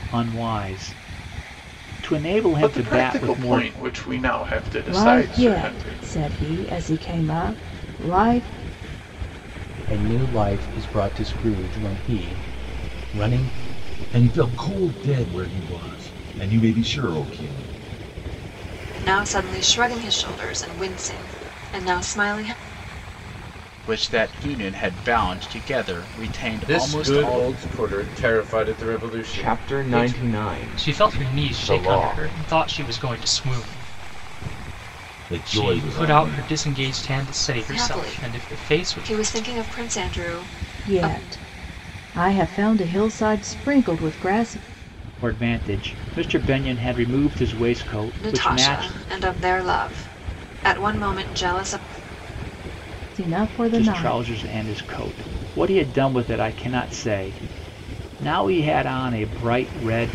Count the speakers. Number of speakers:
10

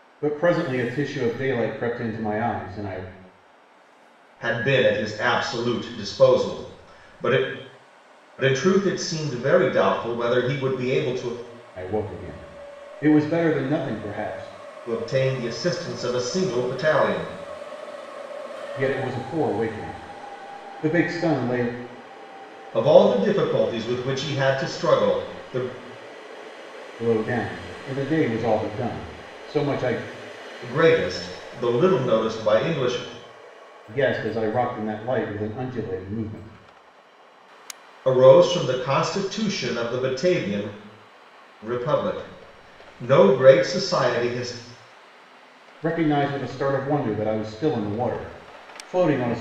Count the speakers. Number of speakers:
2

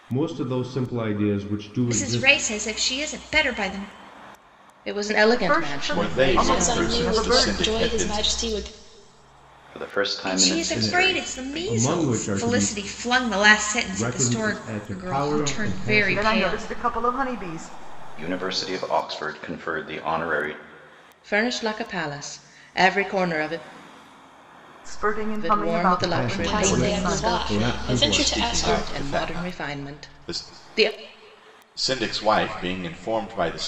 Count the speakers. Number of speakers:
7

